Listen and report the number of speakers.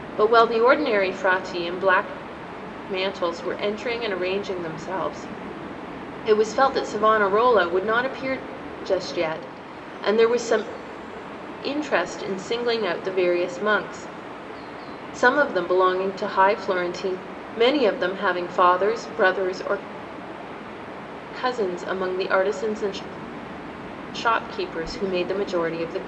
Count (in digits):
1